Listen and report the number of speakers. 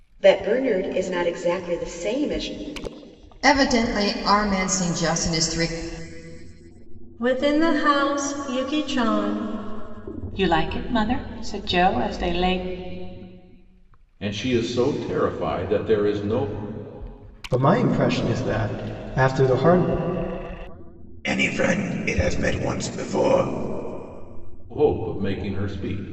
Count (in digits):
7